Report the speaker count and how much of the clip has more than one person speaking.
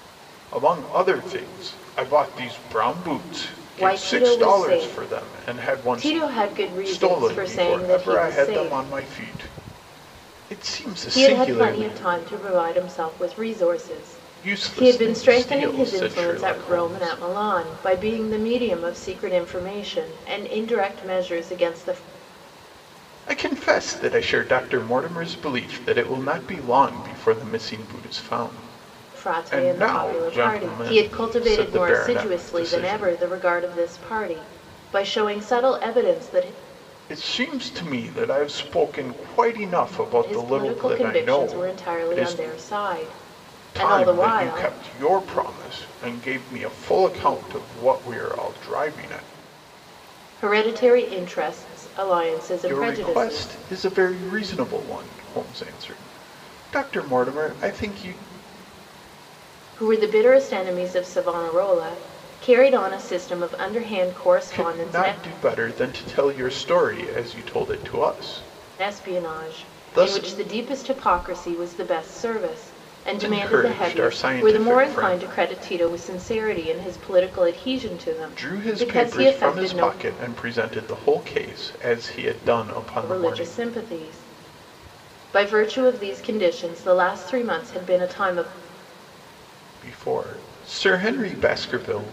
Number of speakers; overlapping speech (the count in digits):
2, about 24%